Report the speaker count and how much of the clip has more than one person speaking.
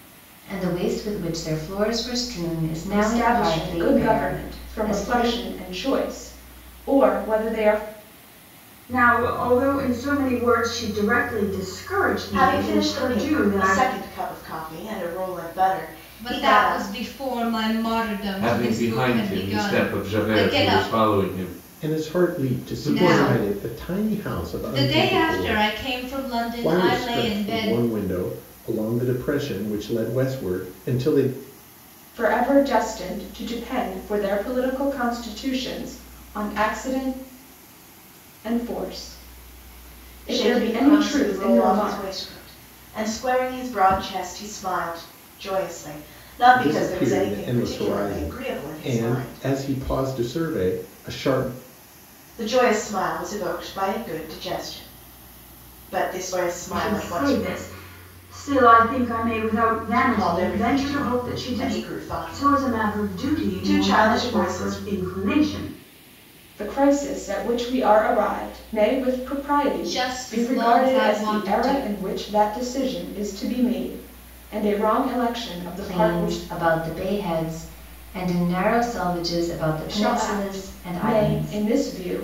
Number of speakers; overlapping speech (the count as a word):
seven, about 33%